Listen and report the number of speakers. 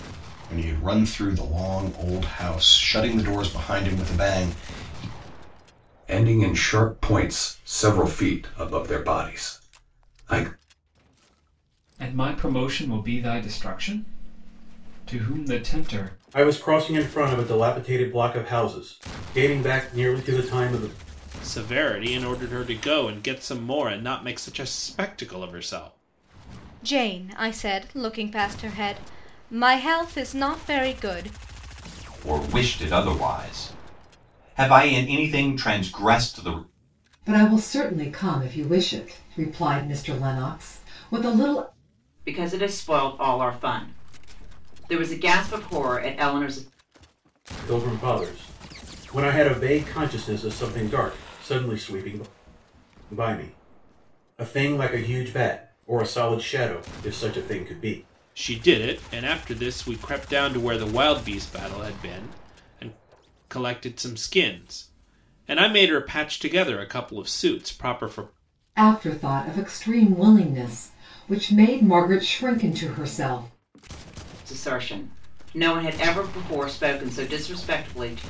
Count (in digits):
9